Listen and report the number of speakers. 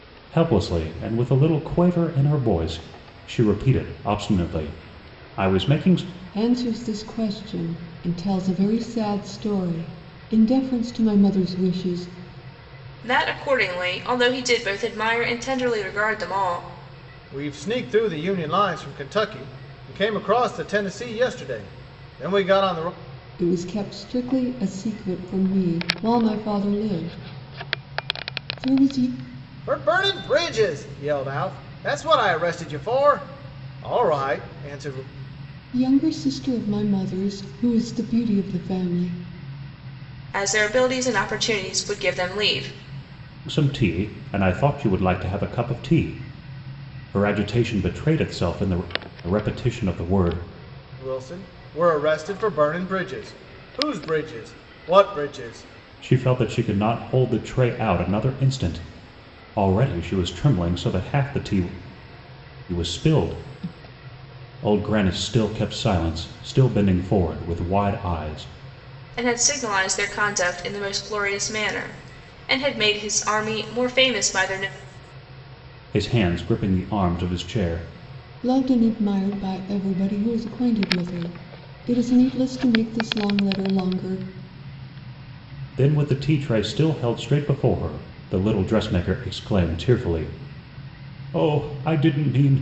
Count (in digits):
4